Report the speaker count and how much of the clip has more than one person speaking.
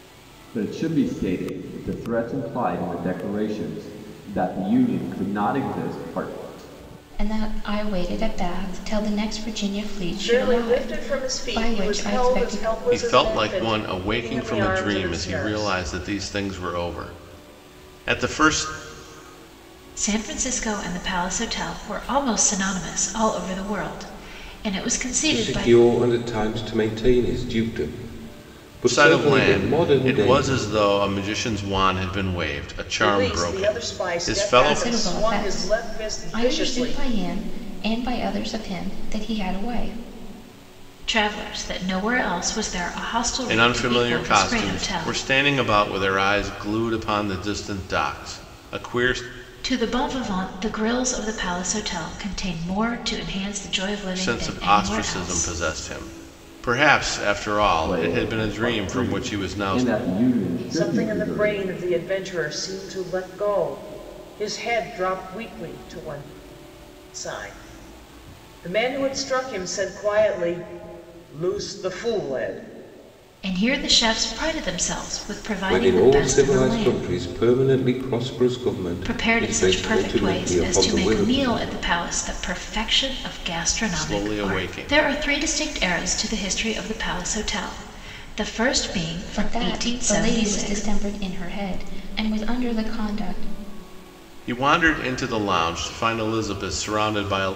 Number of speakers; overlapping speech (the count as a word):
six, about 26%